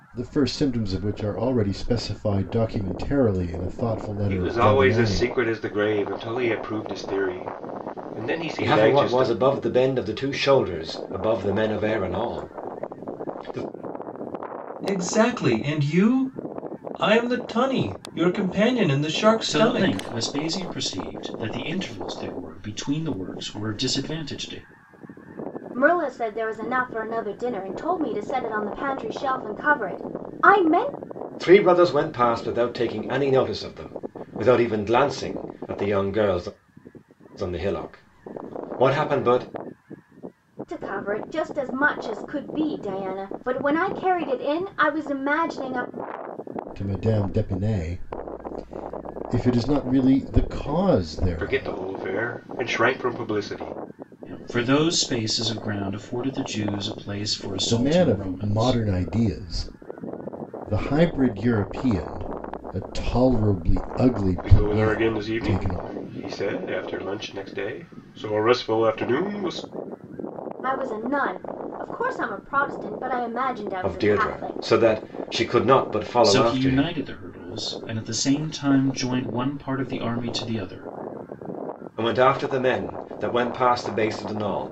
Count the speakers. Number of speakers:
6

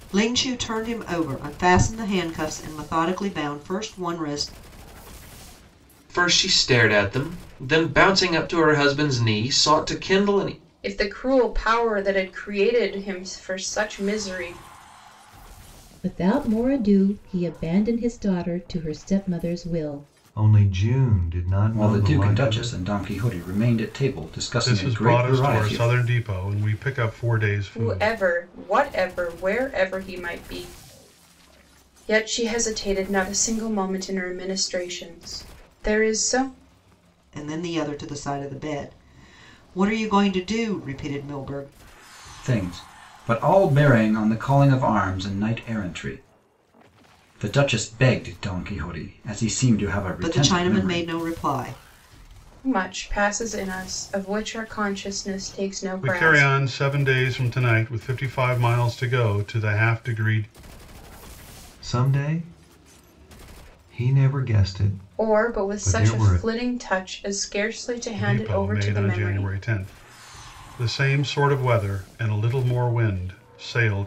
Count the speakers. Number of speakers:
7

